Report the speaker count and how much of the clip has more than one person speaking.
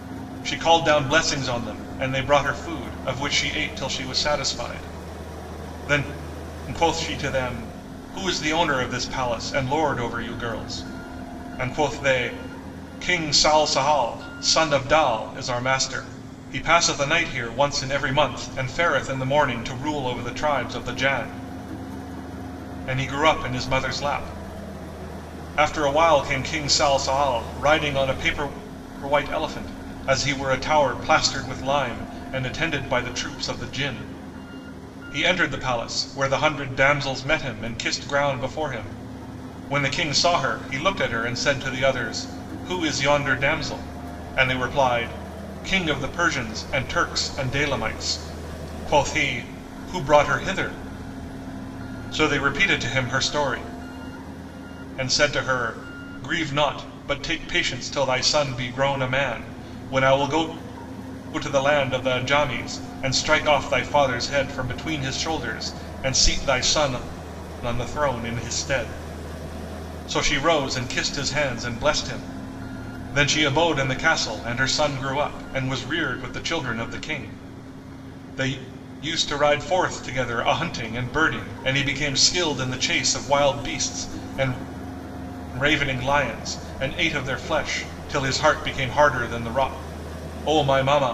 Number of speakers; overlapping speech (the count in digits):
1, no overlap